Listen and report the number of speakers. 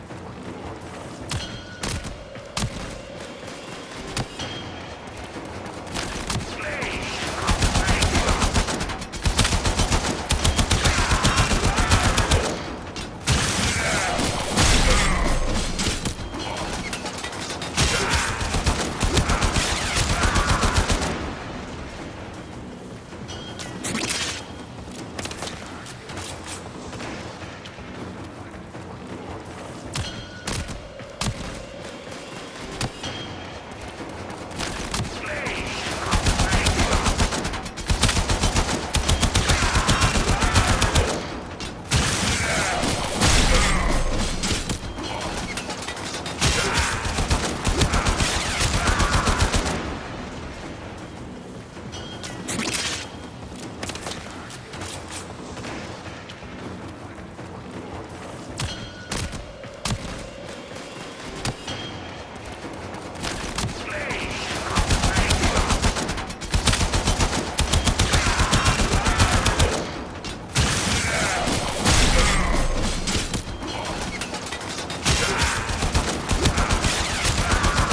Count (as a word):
zero